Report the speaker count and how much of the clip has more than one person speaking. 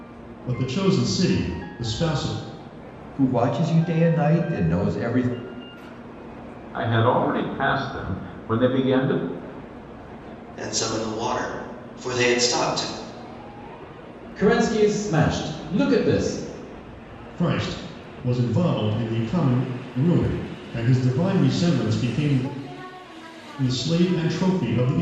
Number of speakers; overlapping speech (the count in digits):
5, no overlap